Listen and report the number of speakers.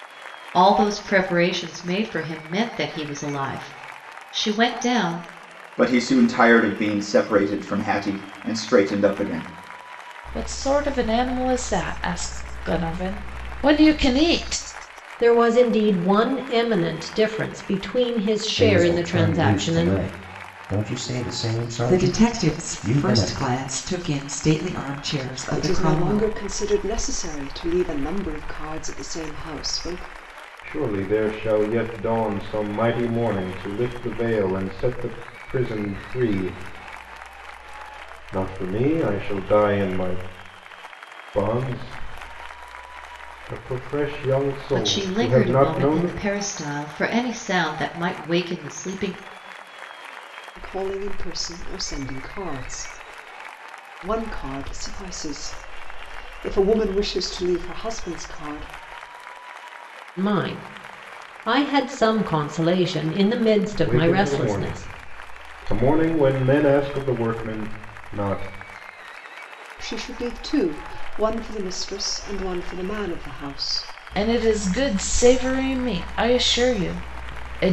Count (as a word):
eight